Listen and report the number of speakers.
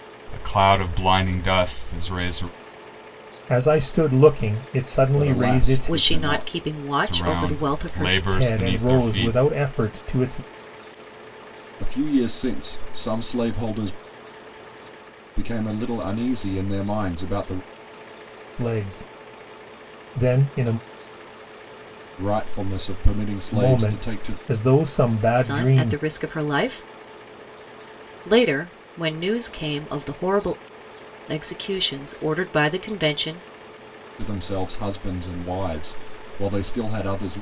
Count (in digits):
4